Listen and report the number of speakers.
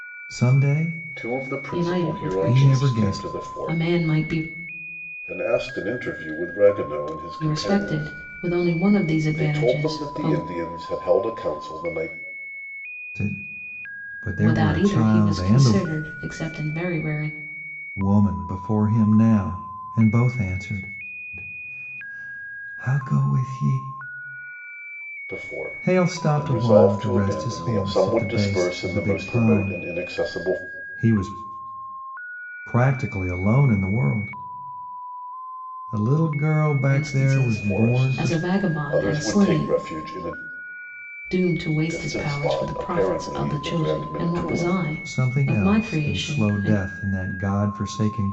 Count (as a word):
three